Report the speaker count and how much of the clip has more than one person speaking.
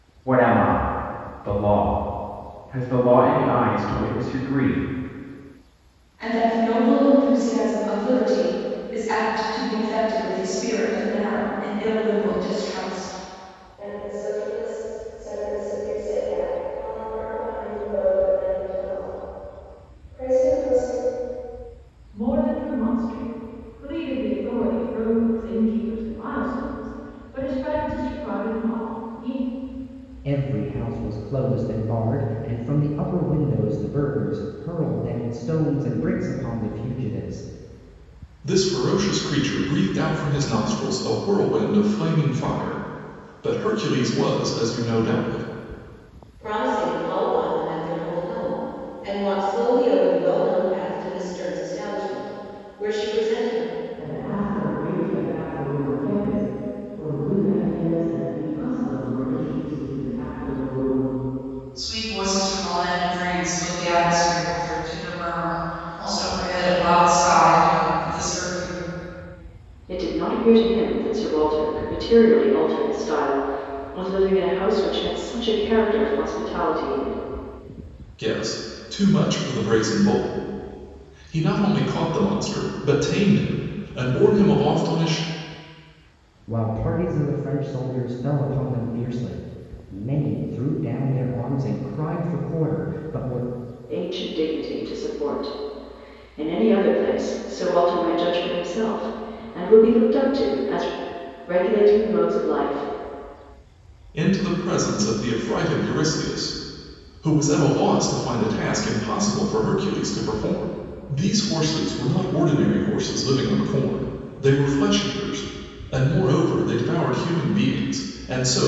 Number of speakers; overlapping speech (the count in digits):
10, no overlap